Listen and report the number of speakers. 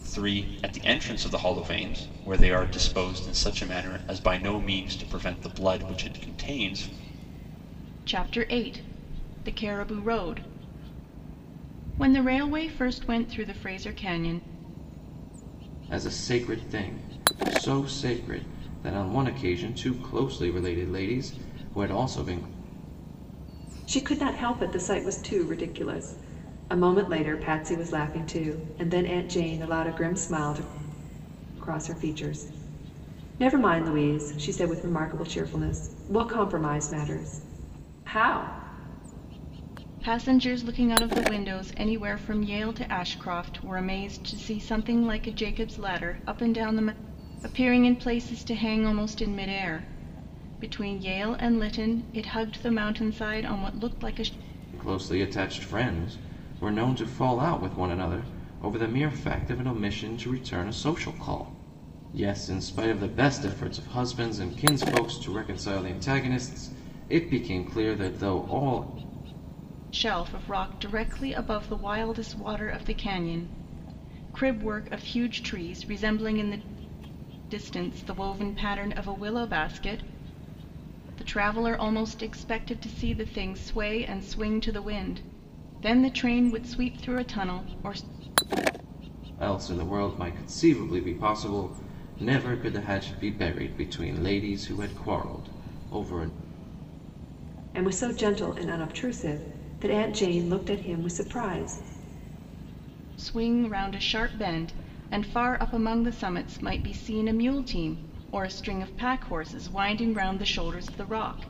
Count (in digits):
4